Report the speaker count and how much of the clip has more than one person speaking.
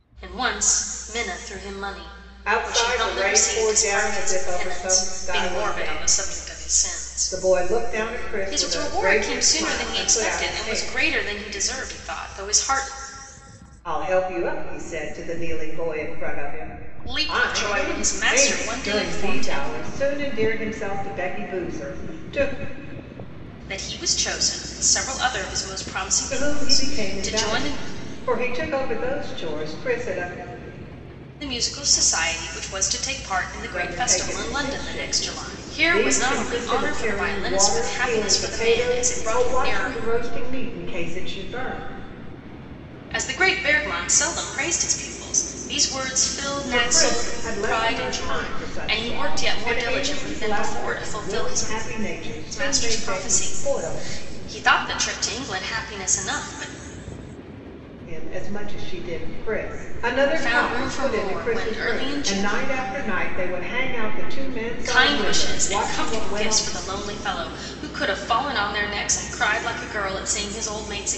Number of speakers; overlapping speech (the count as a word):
two, about 40%